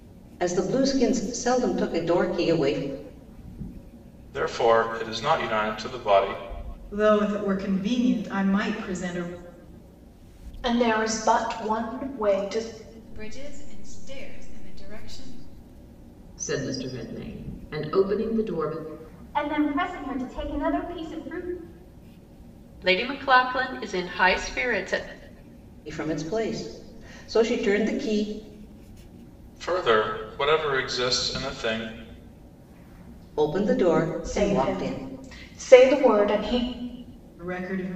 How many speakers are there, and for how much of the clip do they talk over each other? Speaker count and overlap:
8, about 2%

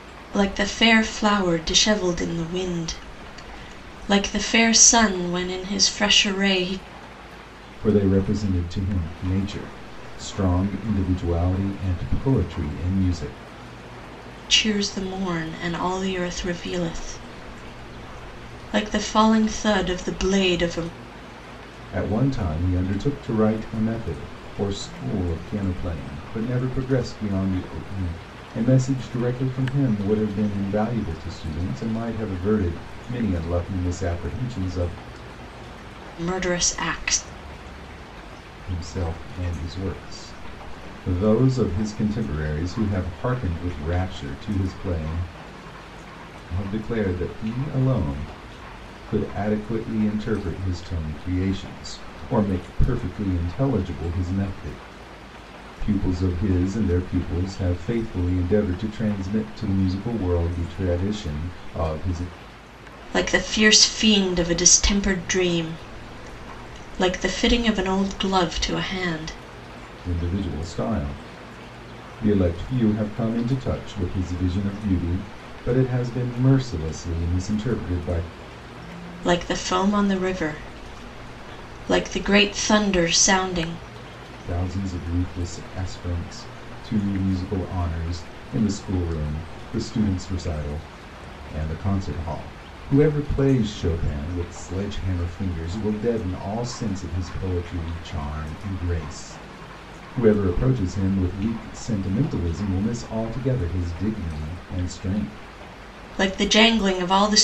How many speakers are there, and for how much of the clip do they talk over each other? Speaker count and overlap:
2, no overlap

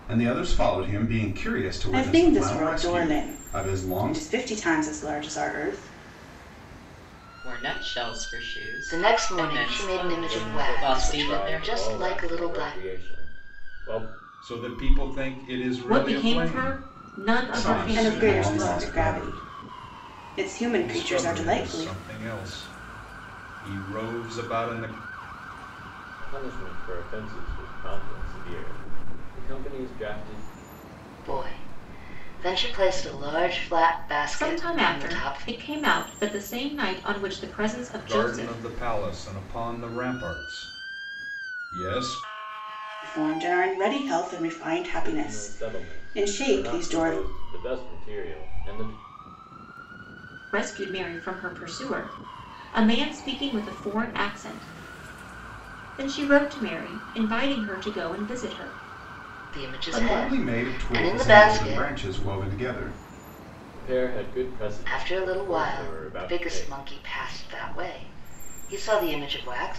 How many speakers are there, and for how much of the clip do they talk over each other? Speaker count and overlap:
7, about 28%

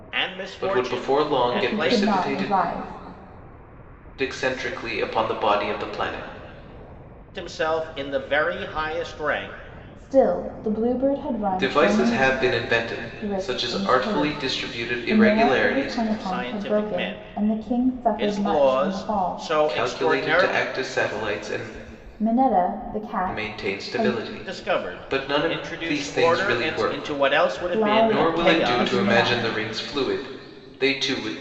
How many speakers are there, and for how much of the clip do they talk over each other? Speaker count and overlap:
3, about 49%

